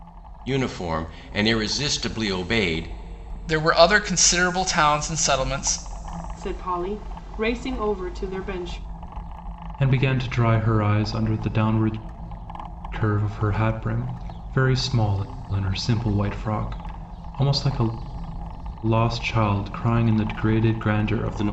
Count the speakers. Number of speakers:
4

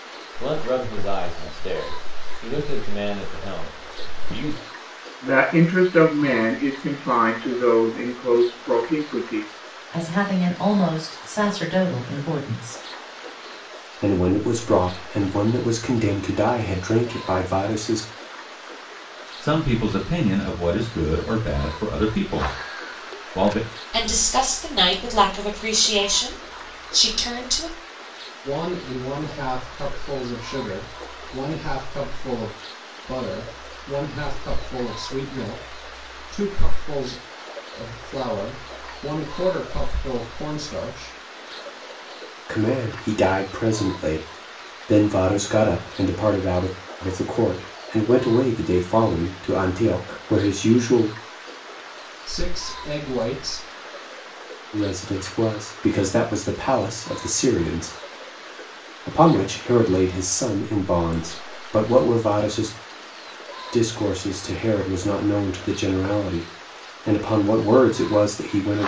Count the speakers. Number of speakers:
7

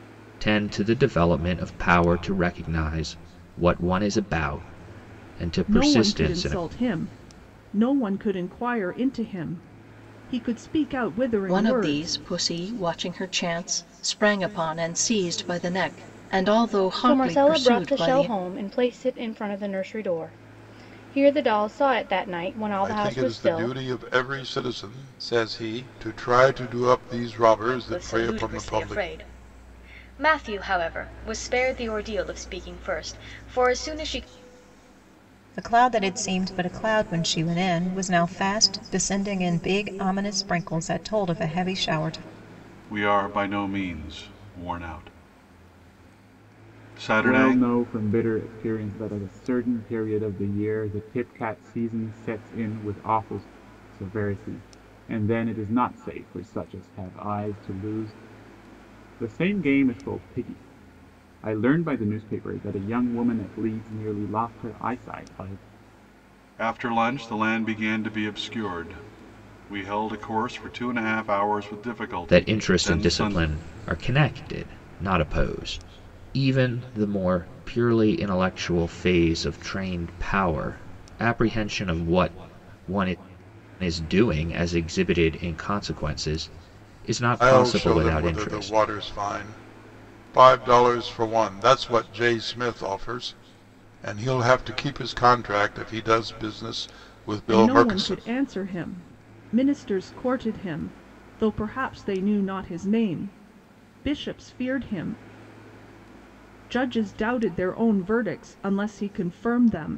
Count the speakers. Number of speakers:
9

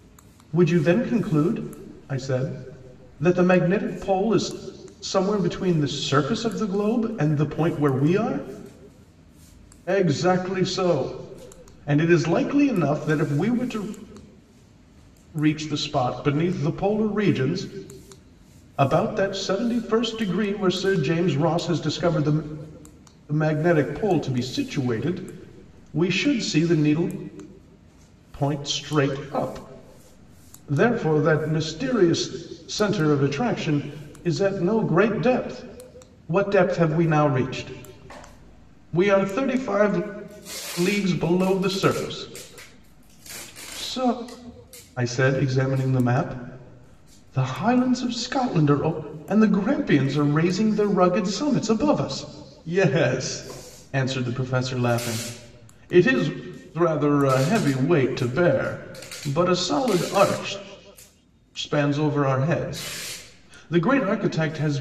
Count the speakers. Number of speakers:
1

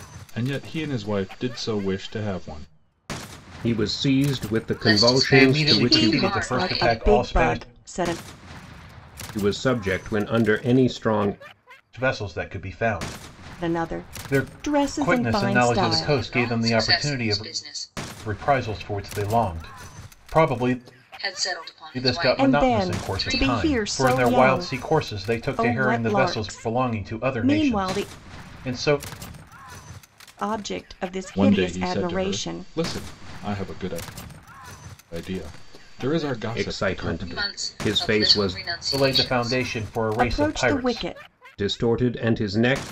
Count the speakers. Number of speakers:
5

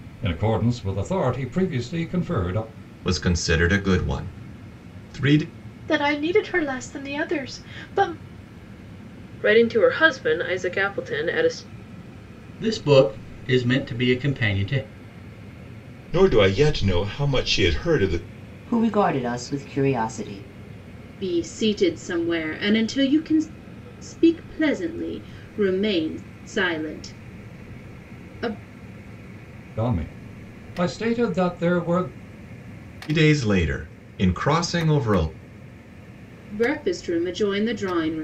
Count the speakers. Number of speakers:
8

